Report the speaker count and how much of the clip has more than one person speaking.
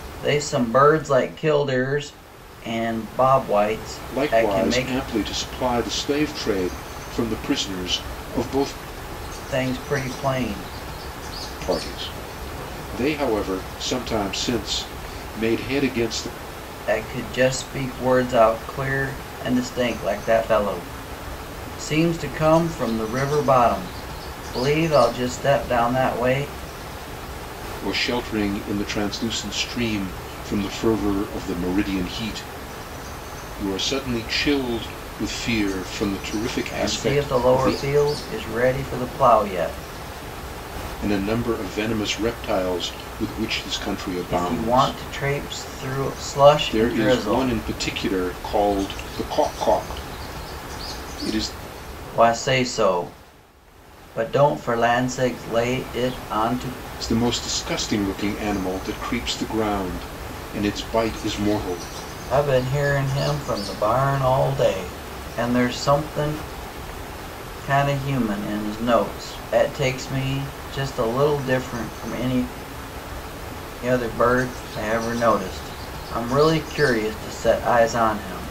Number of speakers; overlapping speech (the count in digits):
2, about 5%